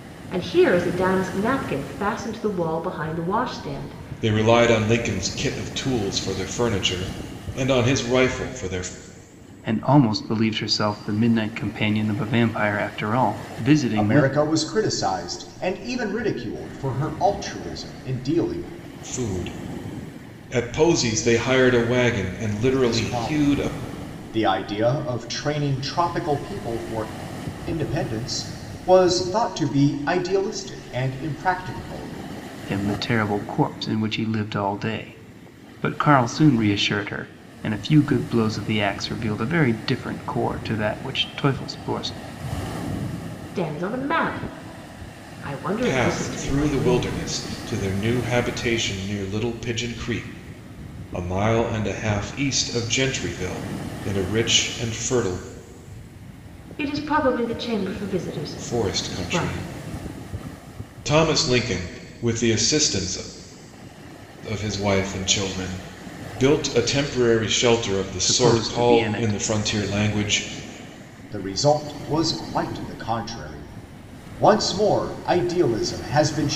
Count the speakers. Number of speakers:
four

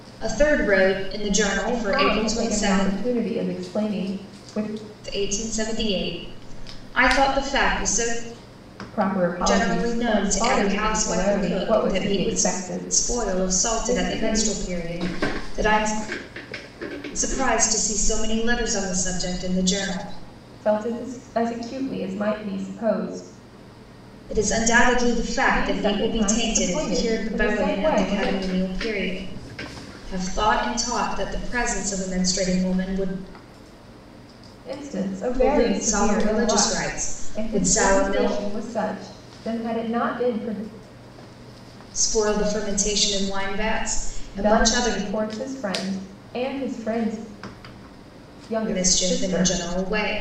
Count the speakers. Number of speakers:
two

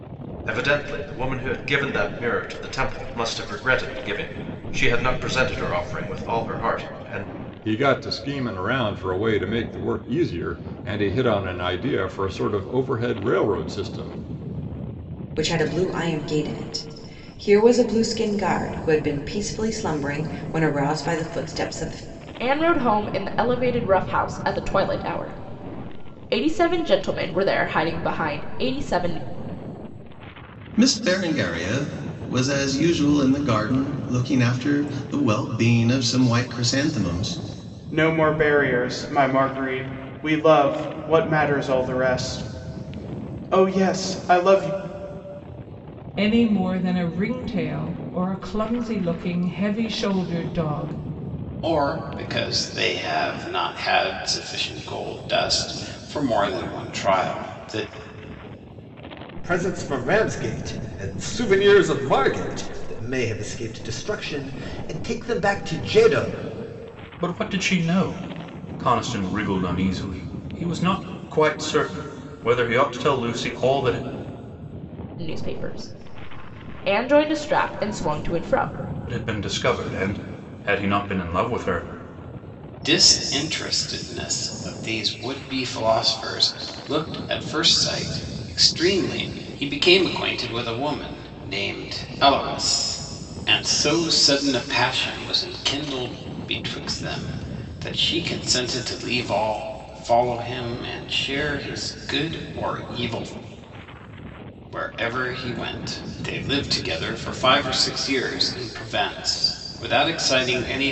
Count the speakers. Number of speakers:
ten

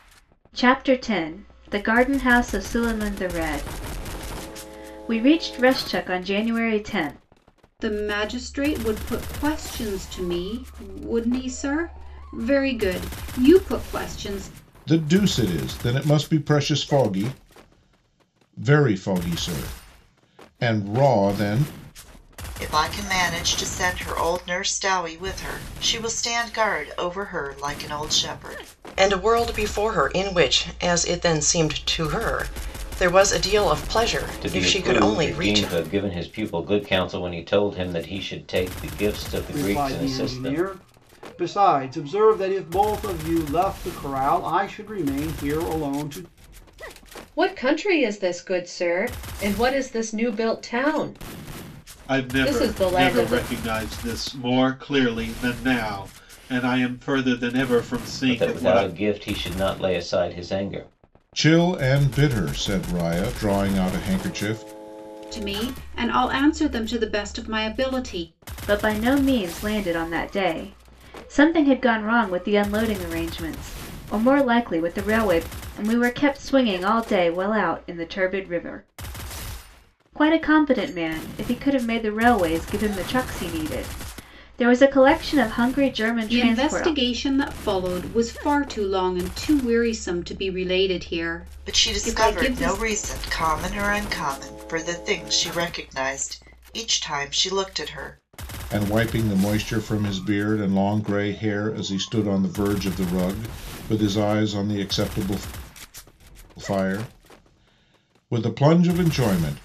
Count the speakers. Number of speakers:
nine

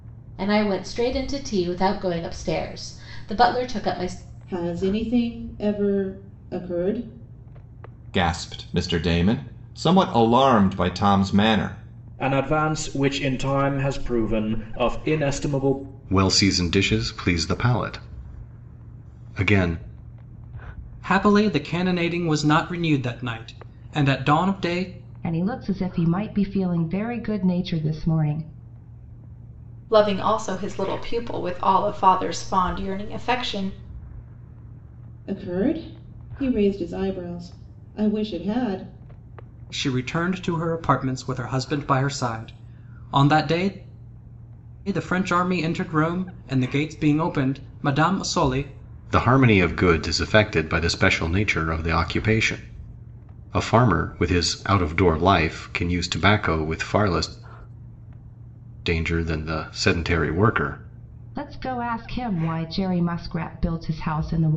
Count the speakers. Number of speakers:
eight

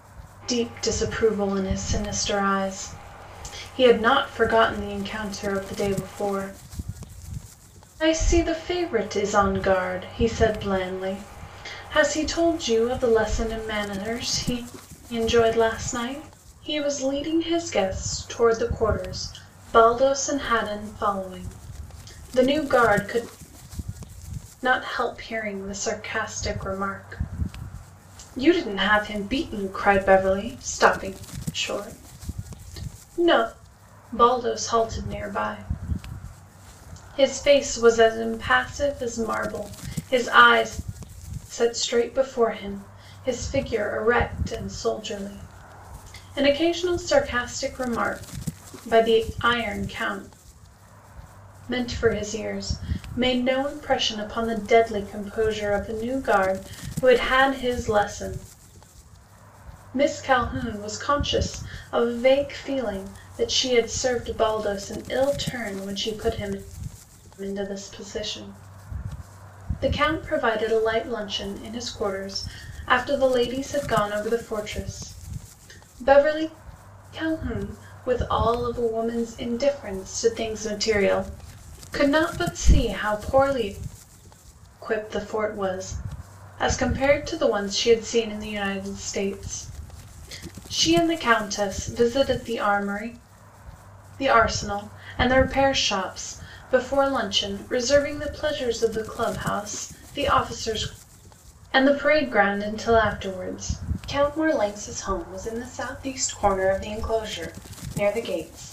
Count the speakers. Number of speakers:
one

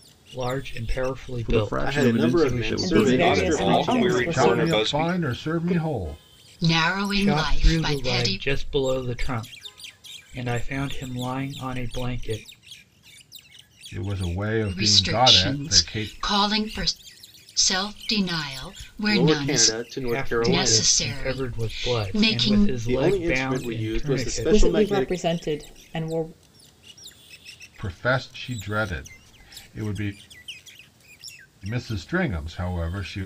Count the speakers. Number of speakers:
eight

